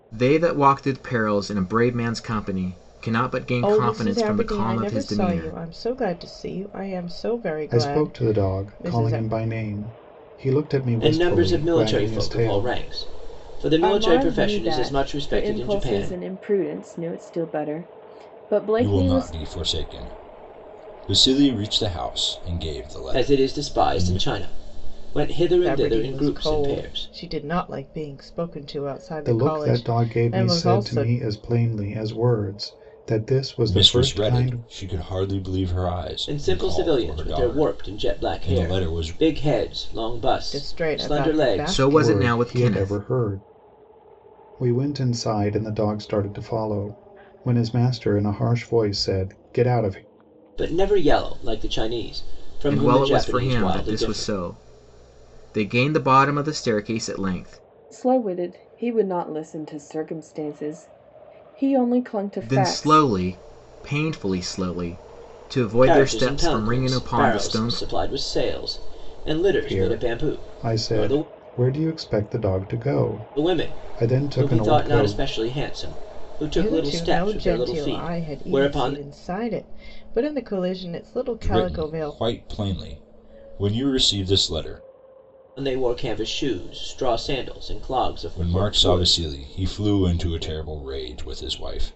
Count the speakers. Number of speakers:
6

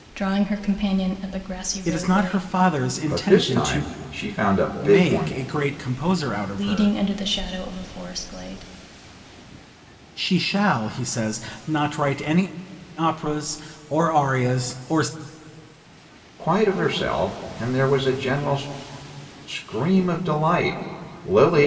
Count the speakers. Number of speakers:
3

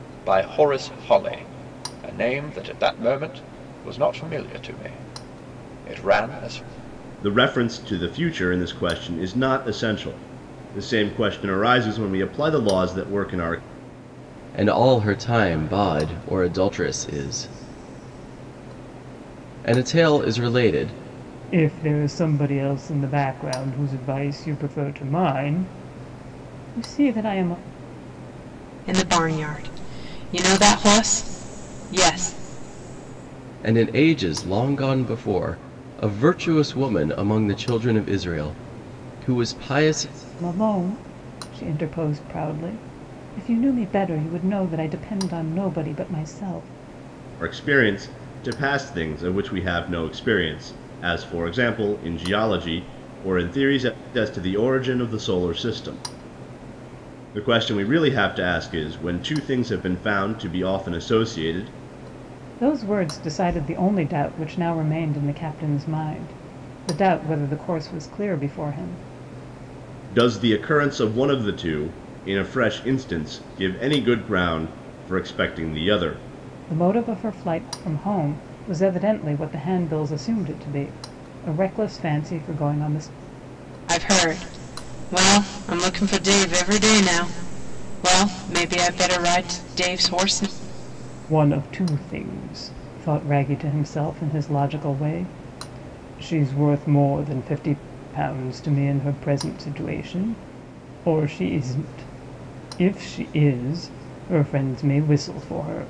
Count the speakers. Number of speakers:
5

